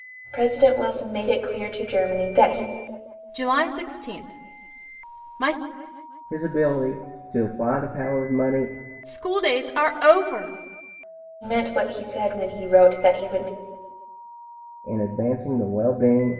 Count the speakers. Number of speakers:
three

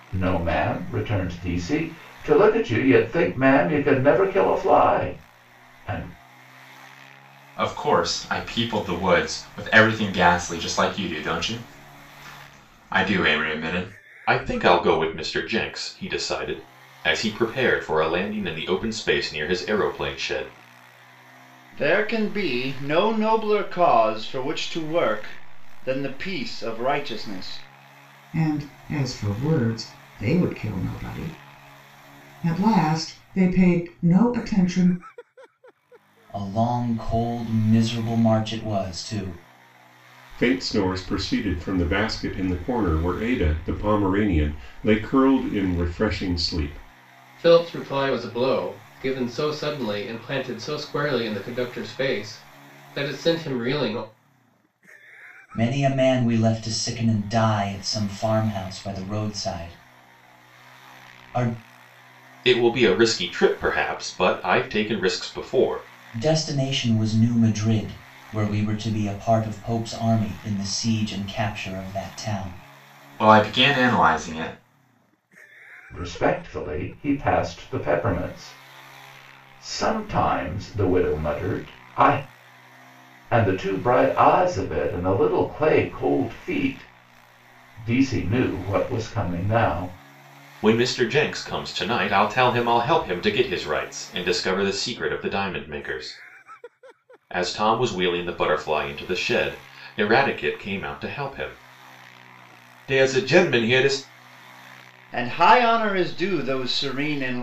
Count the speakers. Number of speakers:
eight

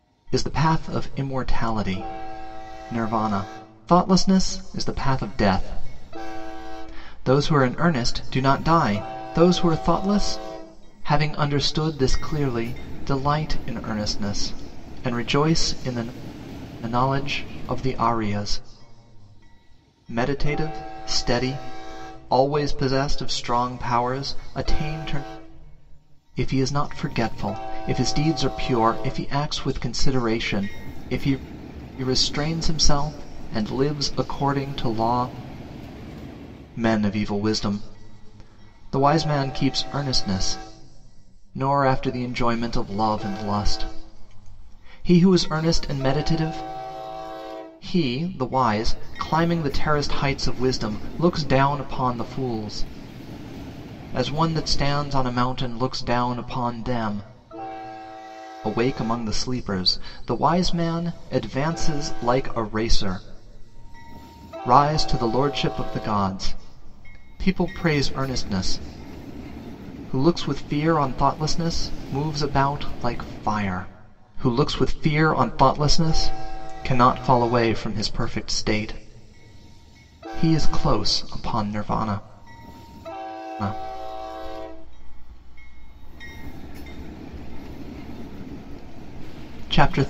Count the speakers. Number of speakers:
one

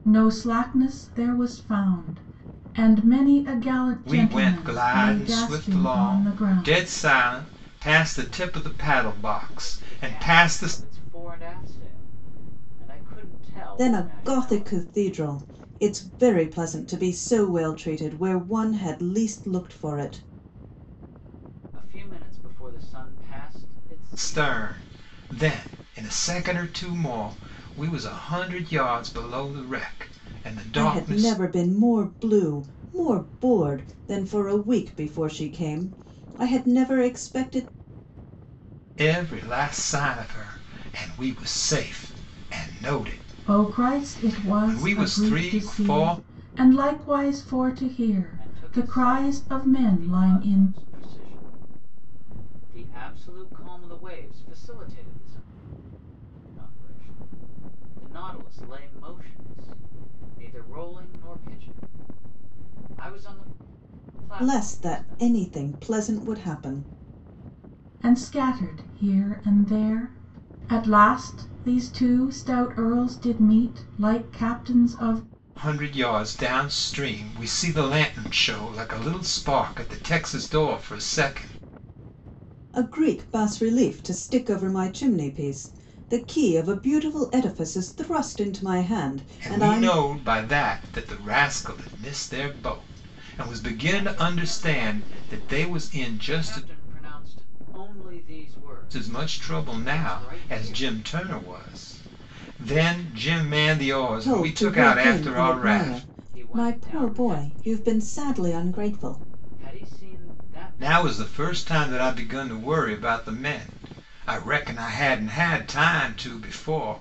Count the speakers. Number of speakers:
four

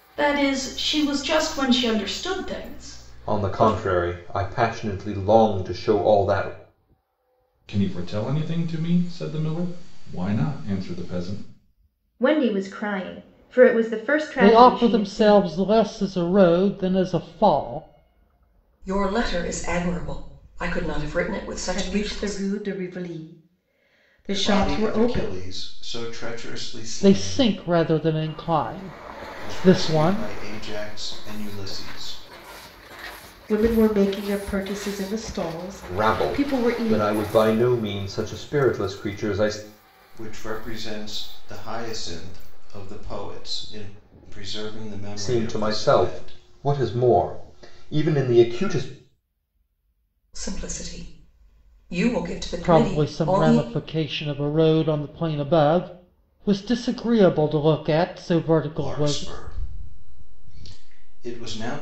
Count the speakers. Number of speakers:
eight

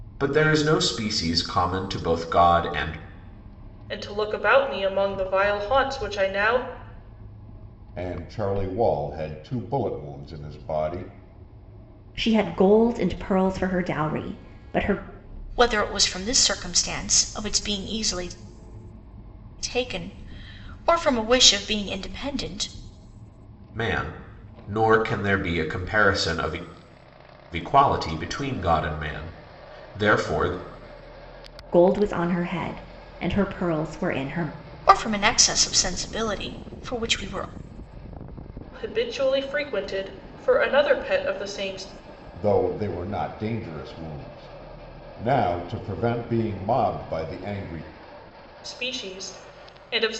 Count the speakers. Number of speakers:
five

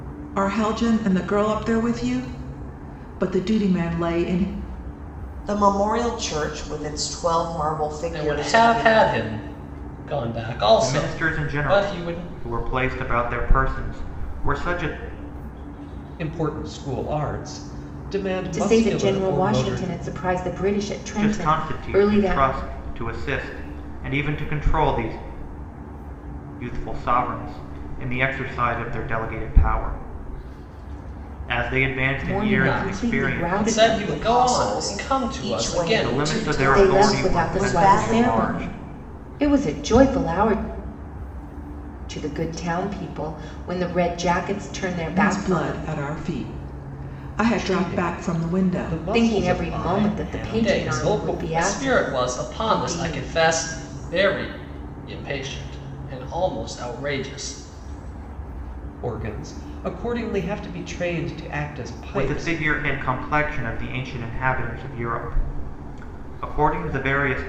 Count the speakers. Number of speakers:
six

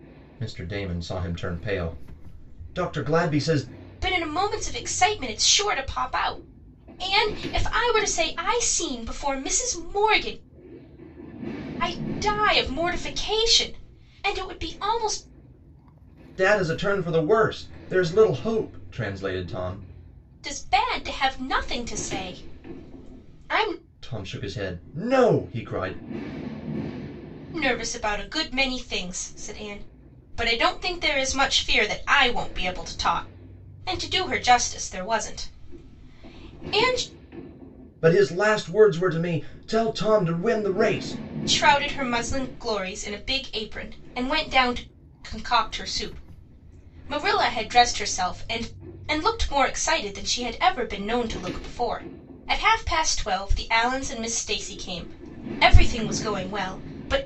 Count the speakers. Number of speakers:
two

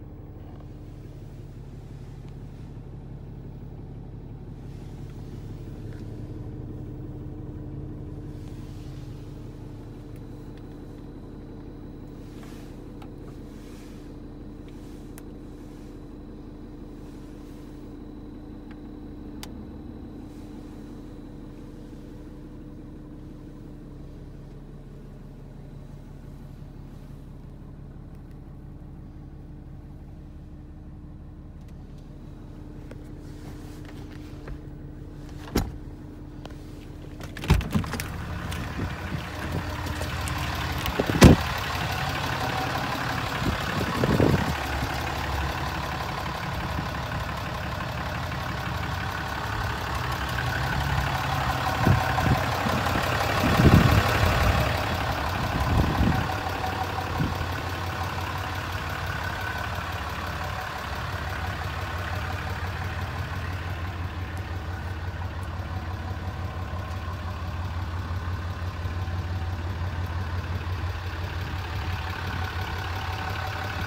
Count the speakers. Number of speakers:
zero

